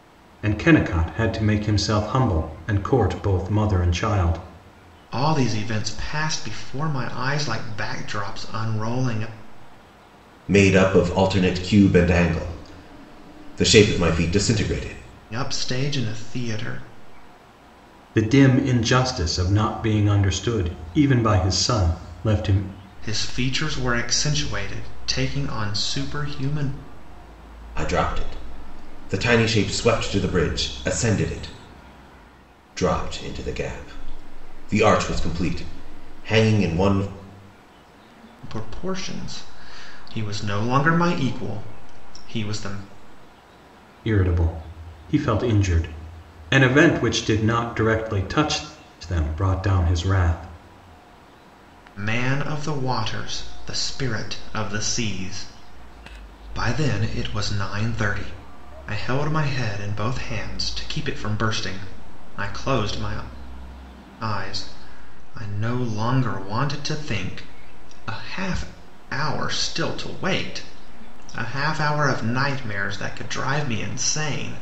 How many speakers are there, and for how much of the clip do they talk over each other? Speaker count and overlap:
3, no overlap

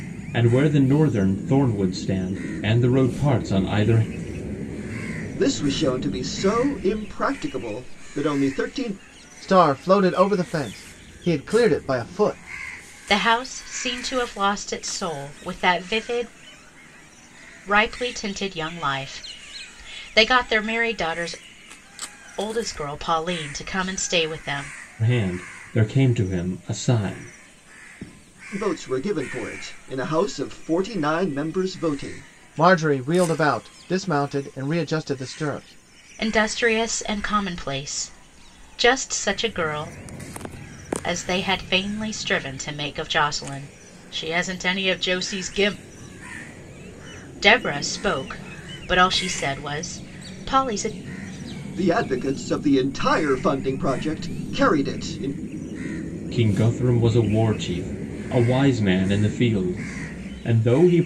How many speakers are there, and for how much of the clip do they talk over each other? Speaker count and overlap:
4, no overlap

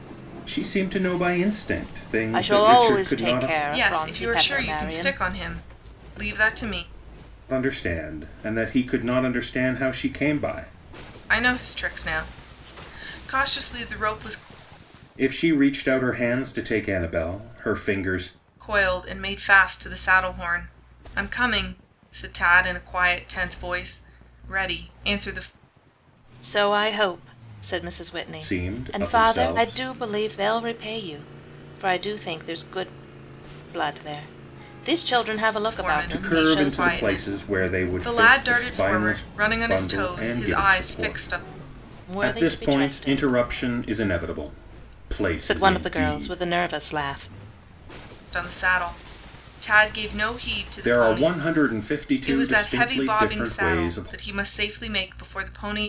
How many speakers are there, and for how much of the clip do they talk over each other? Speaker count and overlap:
3, about 24%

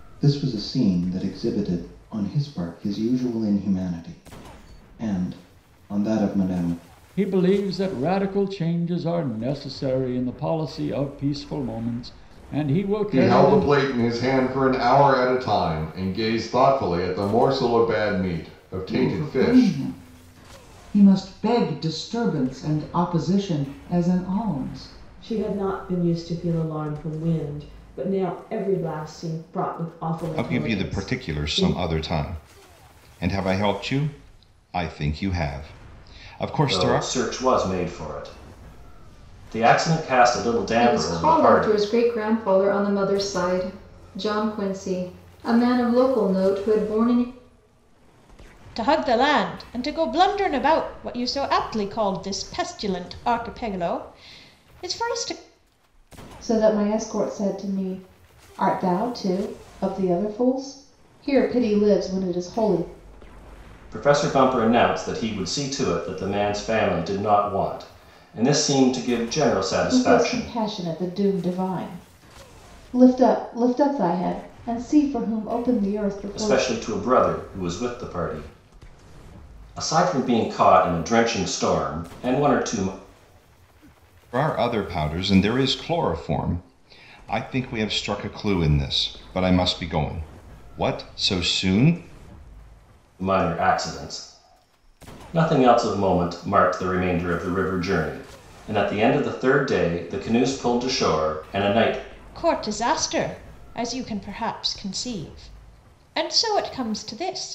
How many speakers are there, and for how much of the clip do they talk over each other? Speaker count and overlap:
10, about 5%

